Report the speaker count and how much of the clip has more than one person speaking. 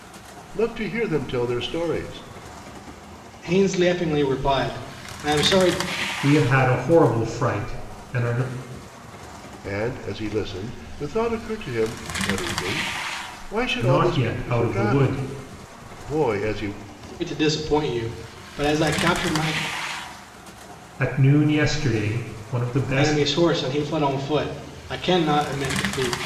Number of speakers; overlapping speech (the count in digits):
3, about 6%